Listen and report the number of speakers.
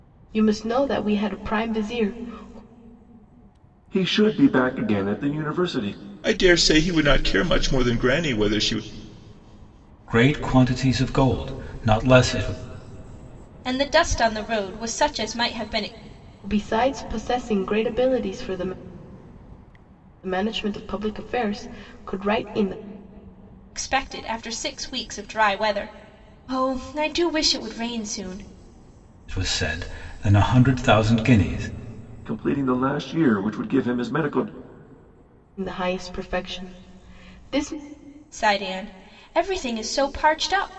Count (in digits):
5